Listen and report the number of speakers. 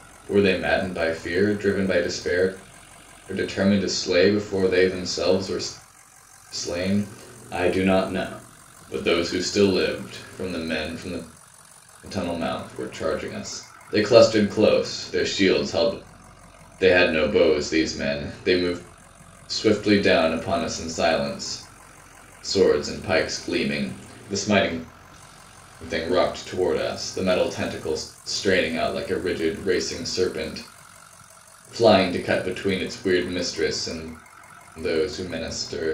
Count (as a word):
one